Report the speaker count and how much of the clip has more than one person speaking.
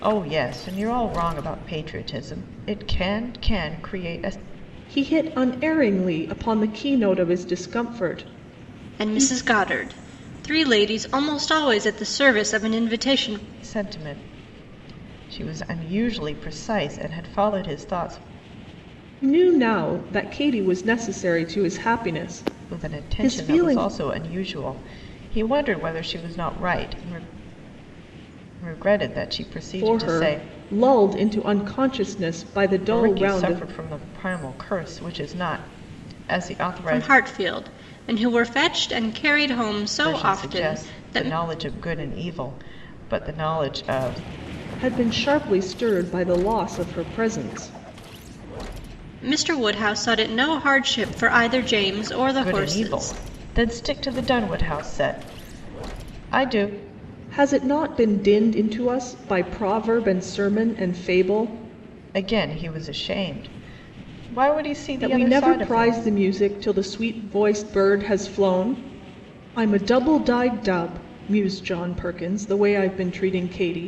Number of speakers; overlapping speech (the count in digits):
3, about 10%